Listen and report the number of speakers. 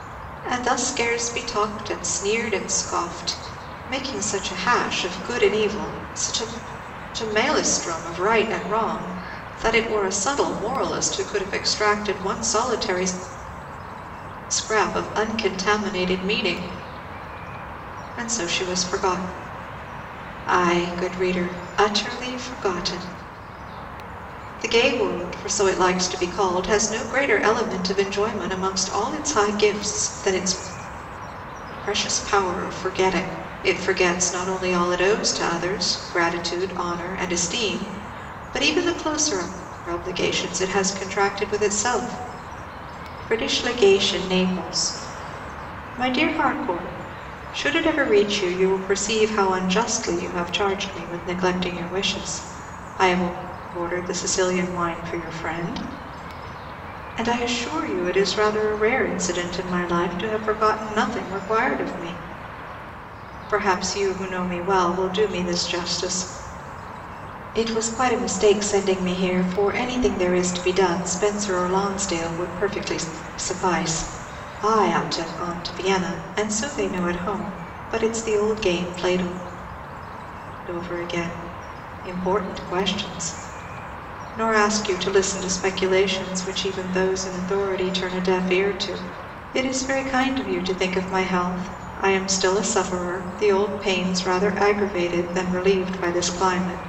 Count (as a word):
one